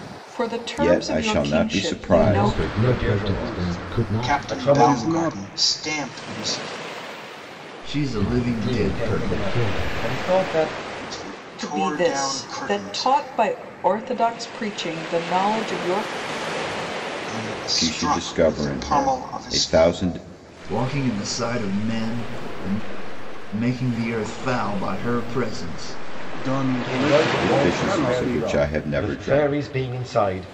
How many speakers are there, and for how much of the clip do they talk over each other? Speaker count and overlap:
7, about 43%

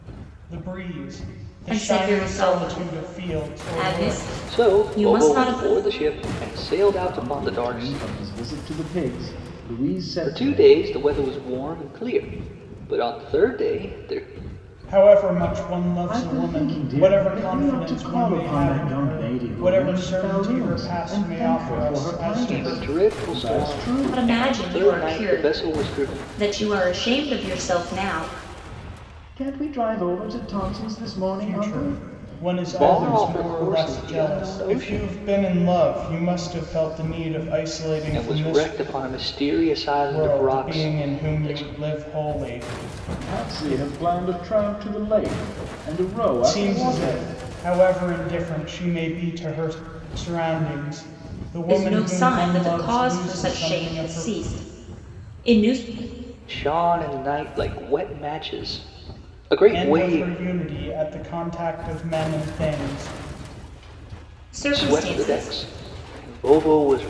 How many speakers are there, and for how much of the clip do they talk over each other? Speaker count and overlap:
4, about 41%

